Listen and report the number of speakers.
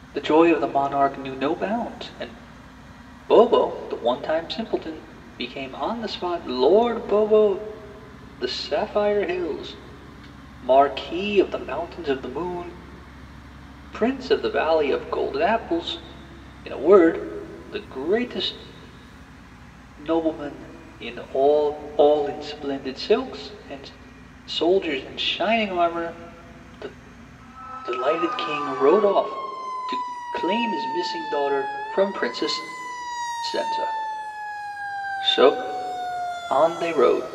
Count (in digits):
1